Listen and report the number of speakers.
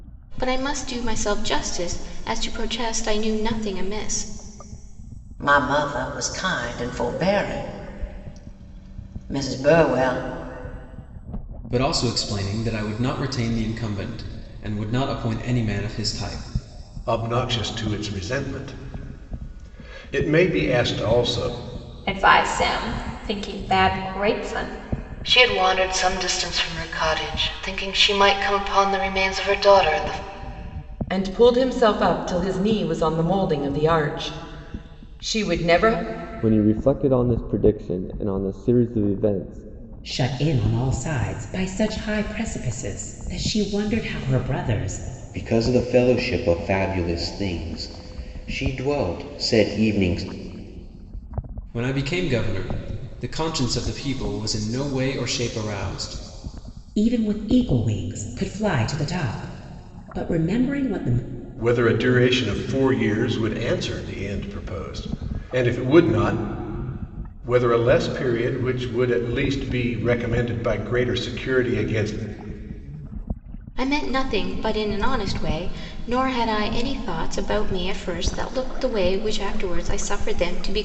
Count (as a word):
ten